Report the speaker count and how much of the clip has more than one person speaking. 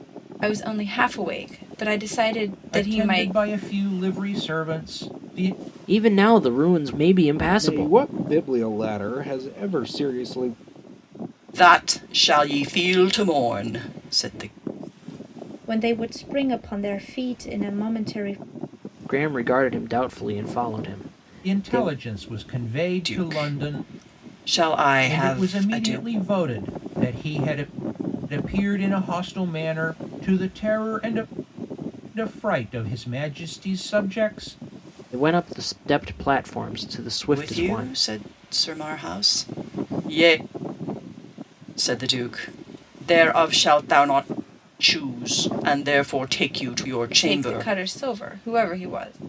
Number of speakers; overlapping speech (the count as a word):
six, about 10%